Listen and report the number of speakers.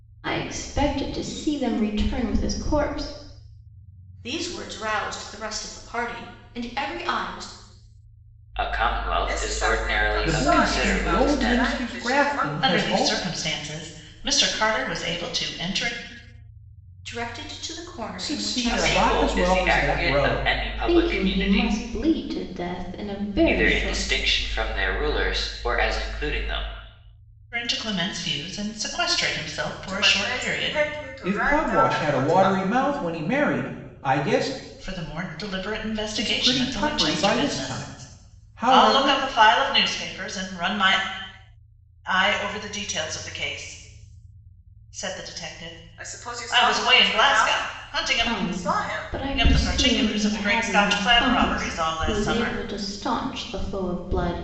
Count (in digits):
6